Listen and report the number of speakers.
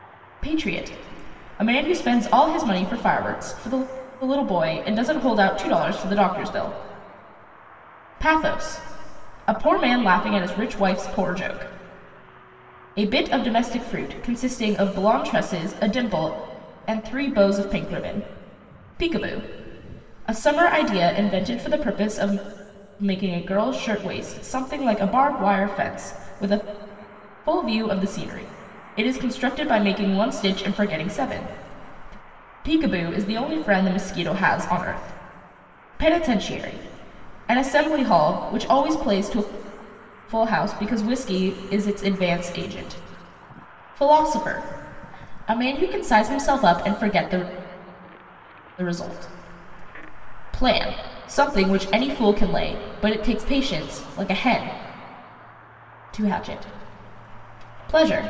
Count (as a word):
one